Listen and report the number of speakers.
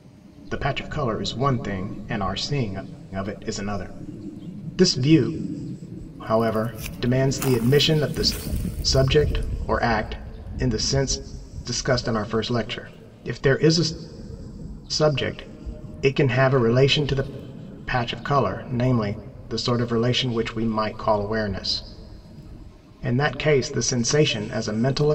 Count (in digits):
1